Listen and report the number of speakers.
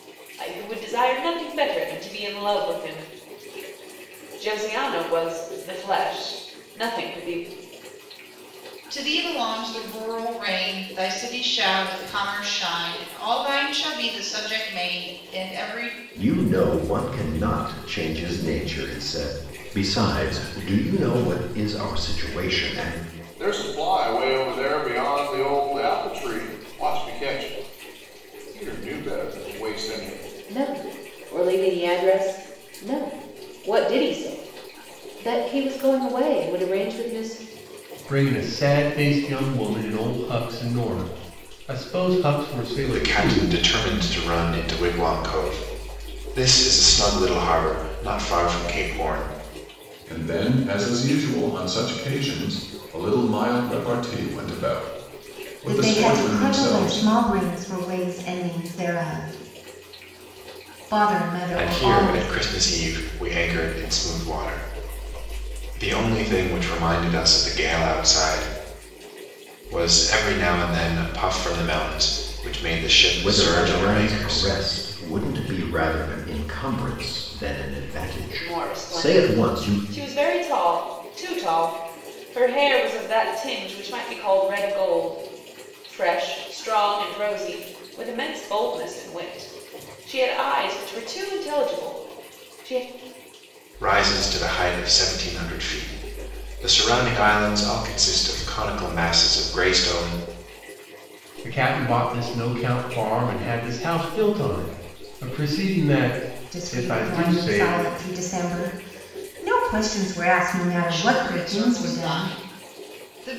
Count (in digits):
9